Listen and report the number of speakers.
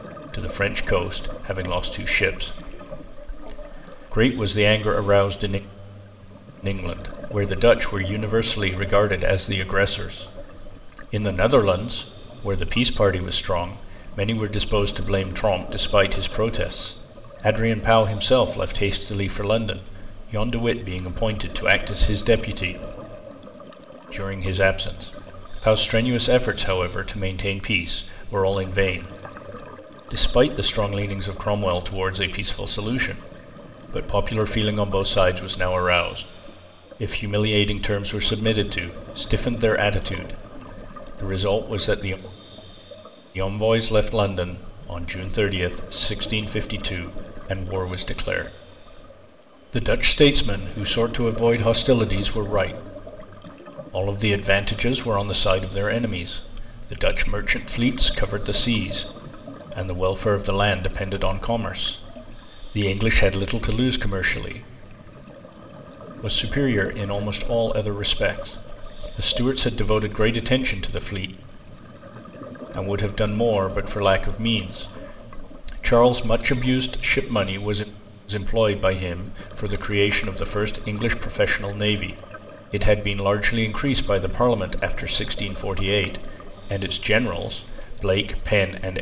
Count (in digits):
1